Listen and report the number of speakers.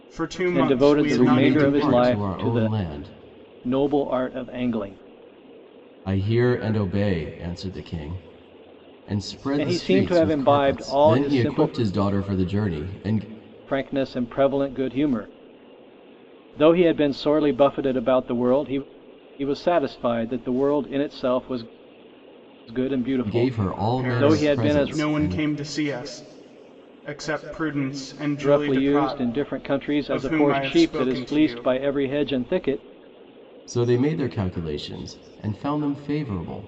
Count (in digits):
3